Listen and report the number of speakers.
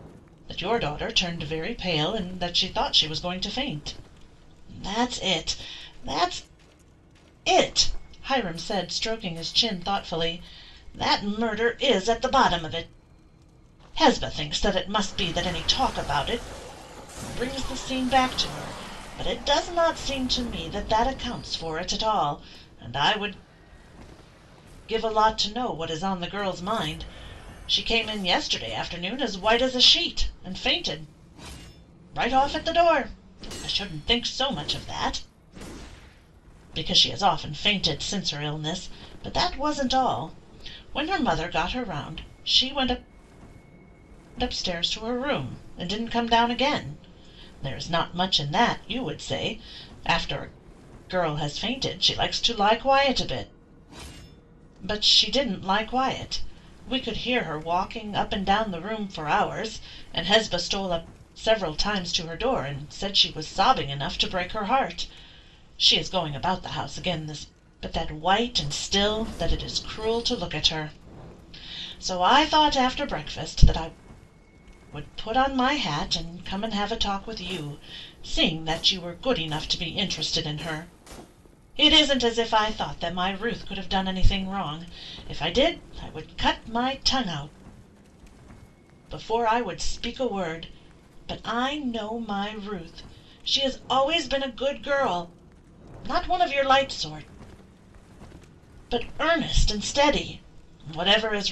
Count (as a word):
one